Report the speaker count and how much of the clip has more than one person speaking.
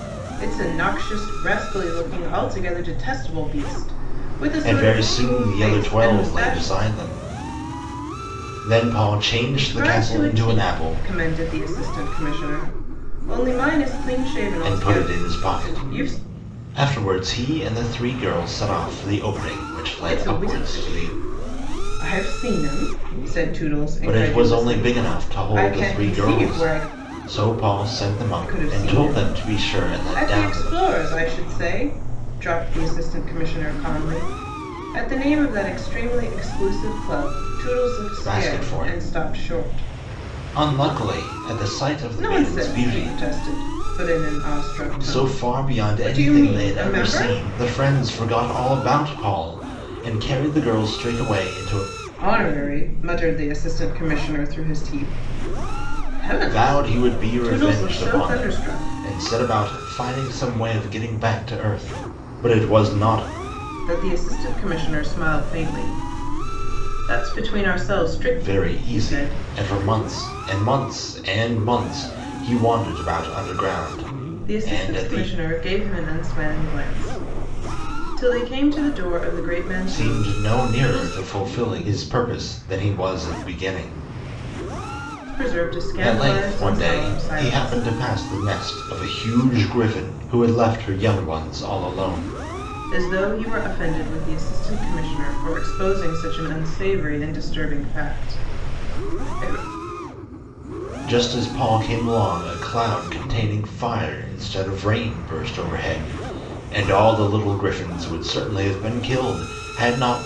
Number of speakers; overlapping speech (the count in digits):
2, about 23%